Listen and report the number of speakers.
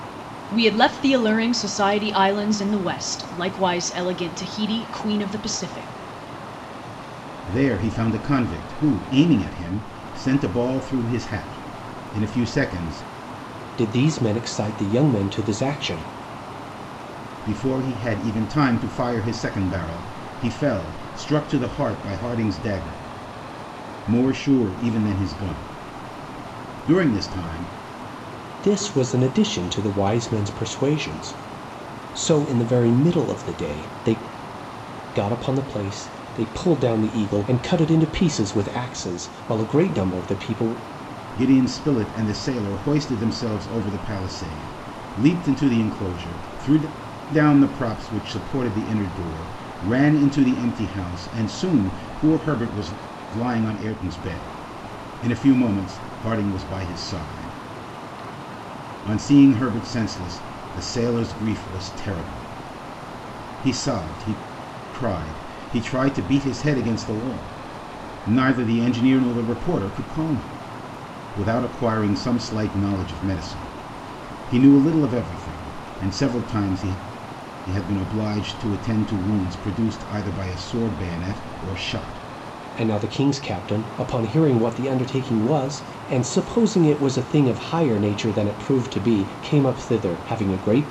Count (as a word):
three